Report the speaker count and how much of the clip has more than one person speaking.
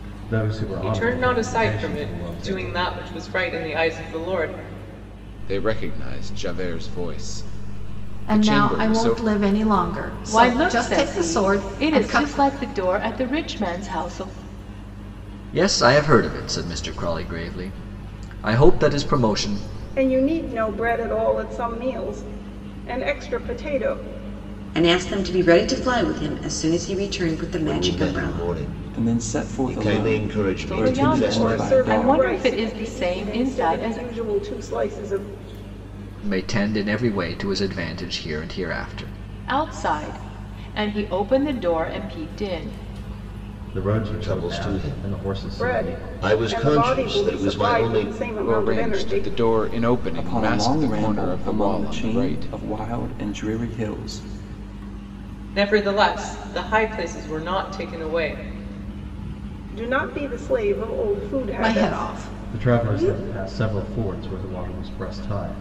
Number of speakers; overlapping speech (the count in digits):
10, about 30%